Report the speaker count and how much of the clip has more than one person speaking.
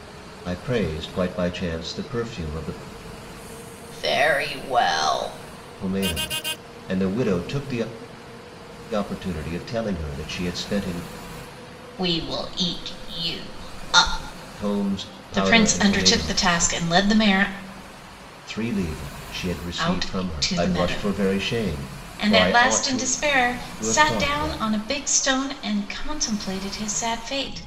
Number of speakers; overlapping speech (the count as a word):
two, about 17%